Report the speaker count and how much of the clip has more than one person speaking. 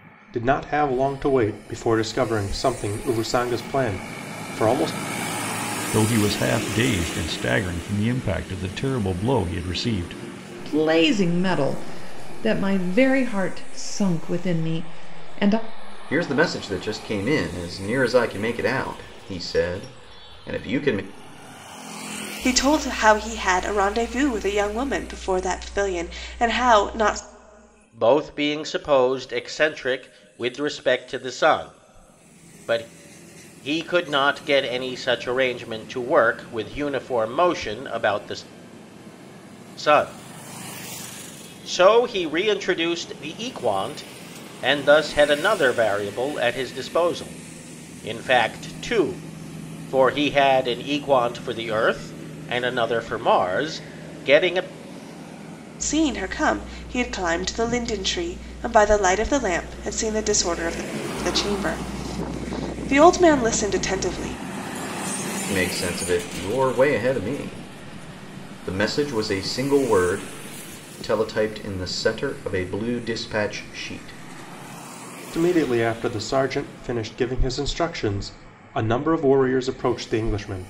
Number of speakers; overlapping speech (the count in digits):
6, no overlap